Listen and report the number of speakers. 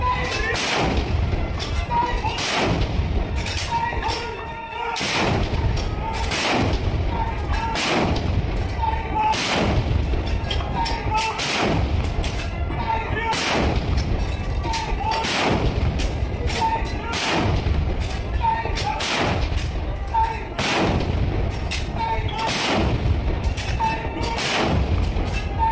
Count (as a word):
zero